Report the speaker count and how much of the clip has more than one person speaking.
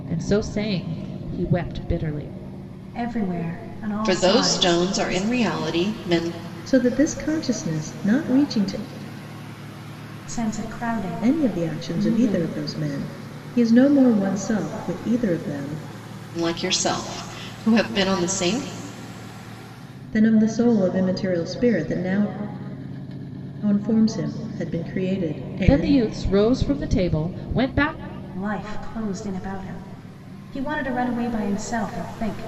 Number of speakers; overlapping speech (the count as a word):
four, about 9%